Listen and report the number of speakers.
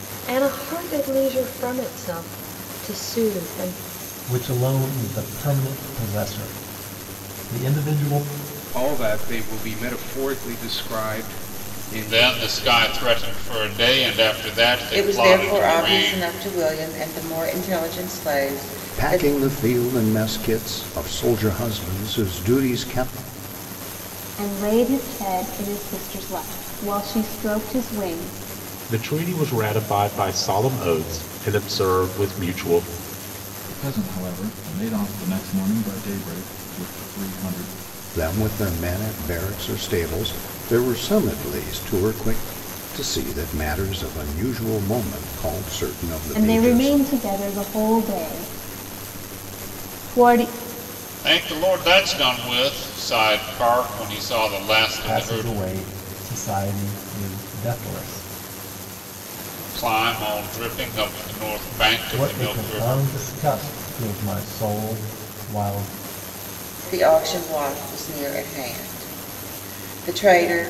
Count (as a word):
nine